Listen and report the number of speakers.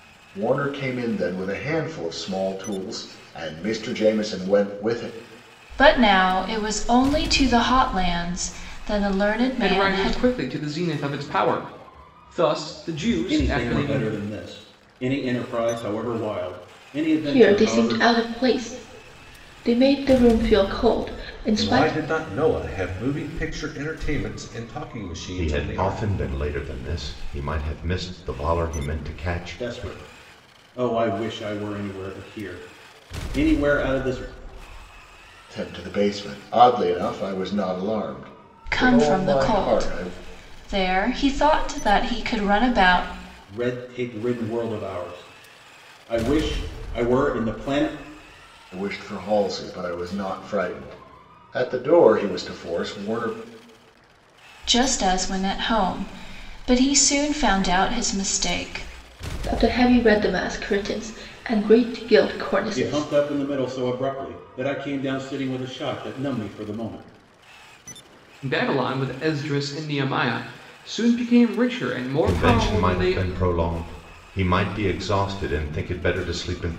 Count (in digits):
7